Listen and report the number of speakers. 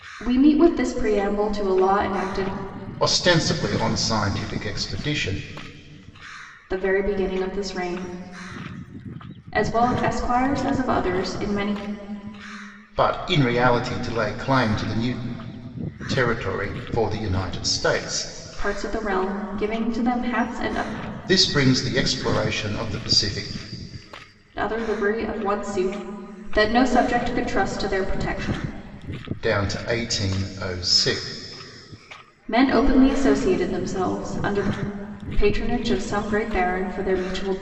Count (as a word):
two